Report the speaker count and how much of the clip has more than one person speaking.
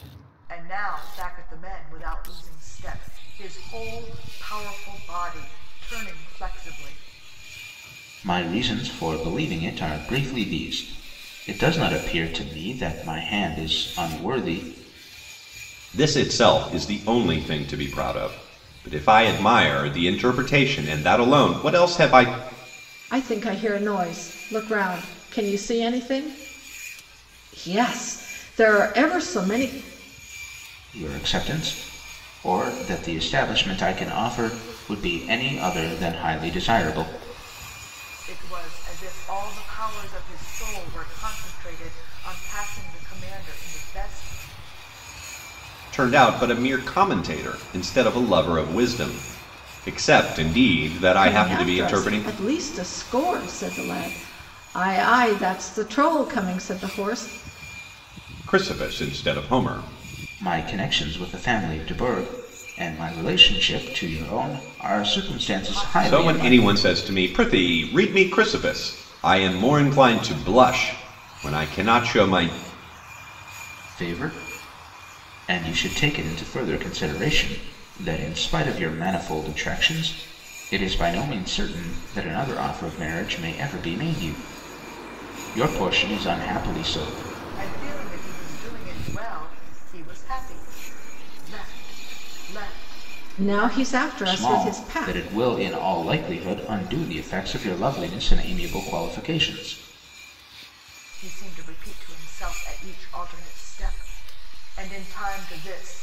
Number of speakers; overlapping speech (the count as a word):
four, about 4%